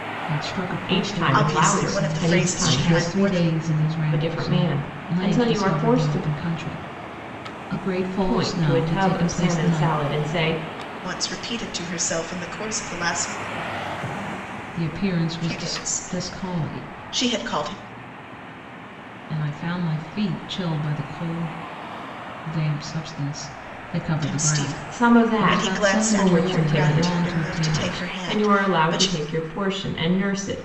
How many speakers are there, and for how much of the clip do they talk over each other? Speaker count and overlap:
3, about 42%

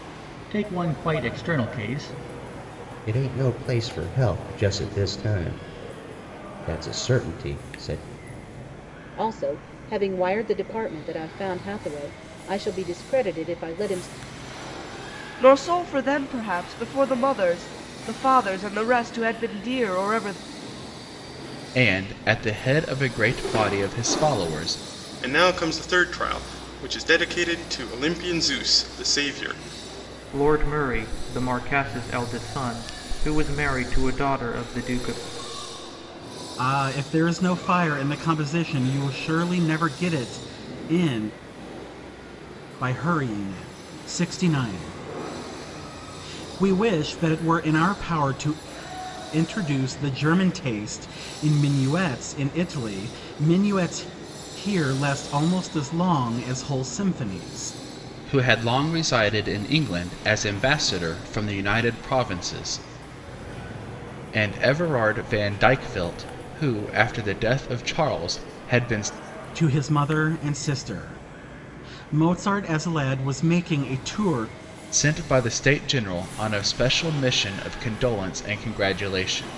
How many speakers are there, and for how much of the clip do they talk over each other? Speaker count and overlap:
8, no overlap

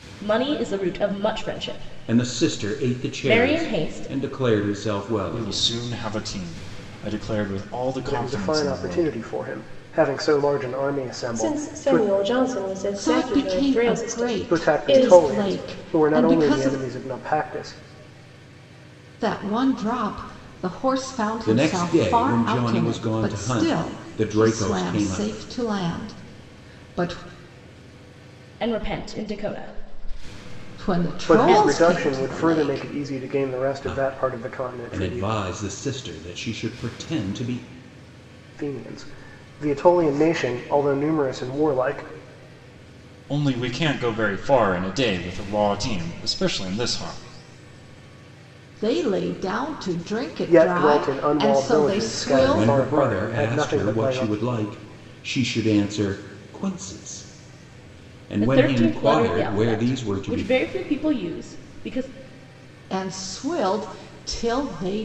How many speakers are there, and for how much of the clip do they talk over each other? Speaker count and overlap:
6, about 34%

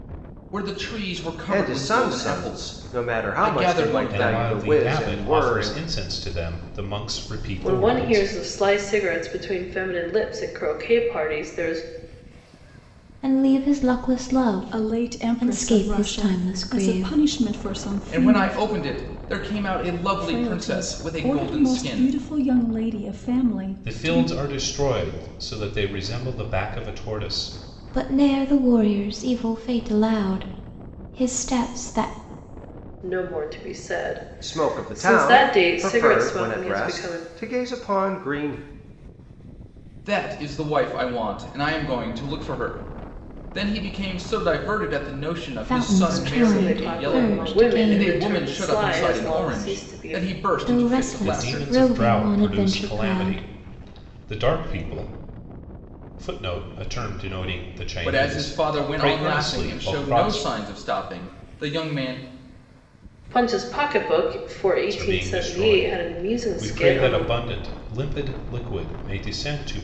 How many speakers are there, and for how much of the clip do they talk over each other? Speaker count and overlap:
6, about 37%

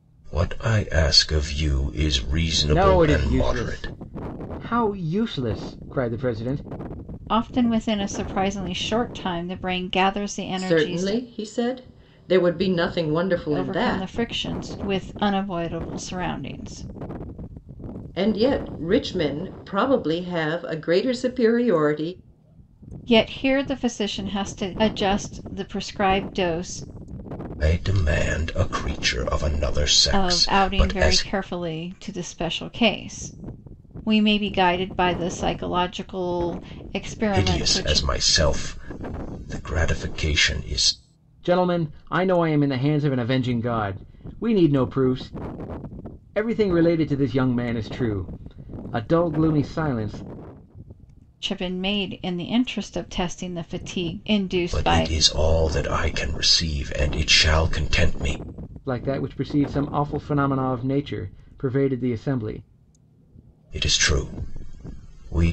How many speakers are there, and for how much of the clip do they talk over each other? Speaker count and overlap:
4, about 8%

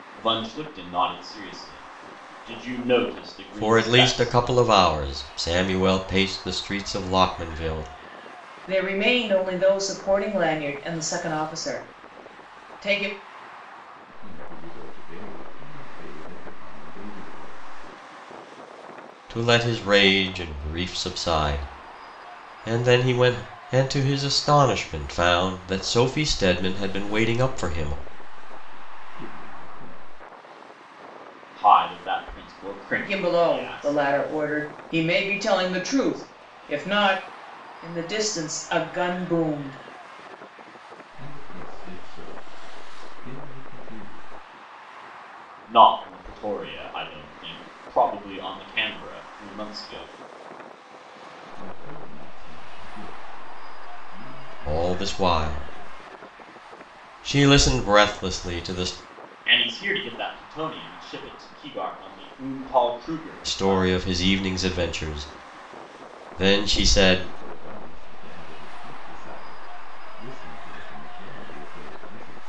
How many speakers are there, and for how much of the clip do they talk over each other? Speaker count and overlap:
4, about 9%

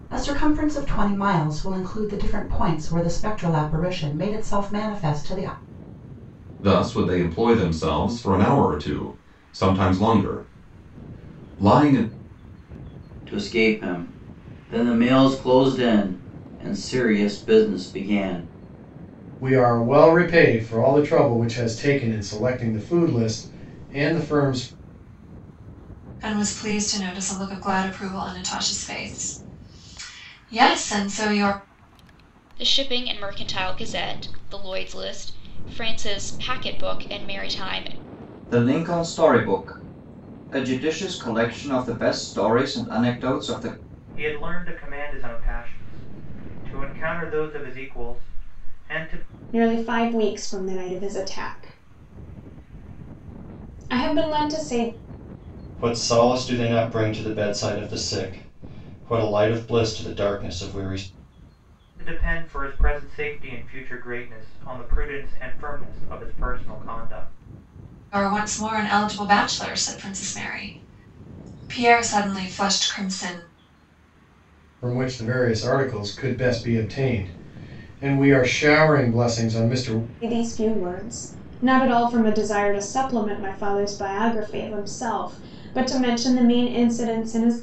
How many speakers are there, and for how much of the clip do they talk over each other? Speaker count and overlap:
10, no overlap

